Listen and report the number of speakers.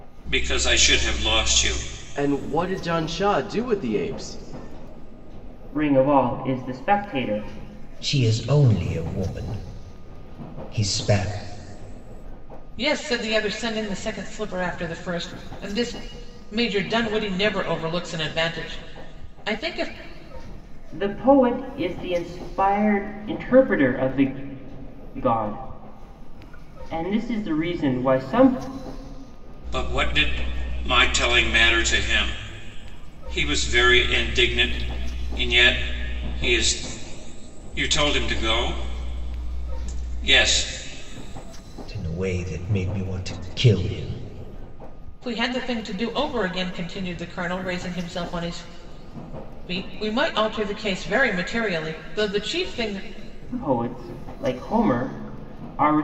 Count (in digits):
5